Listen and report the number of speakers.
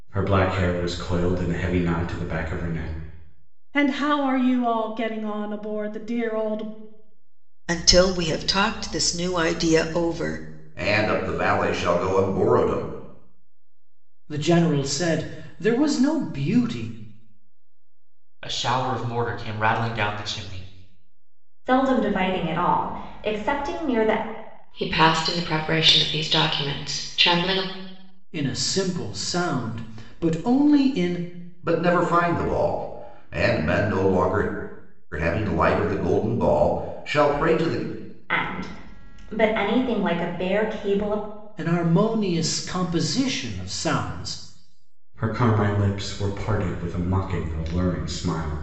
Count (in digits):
8